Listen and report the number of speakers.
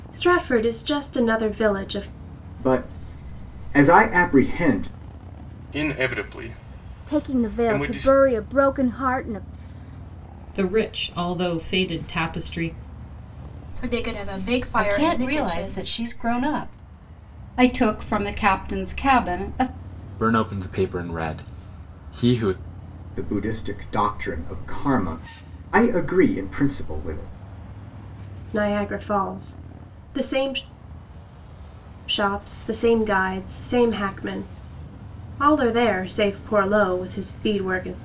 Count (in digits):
9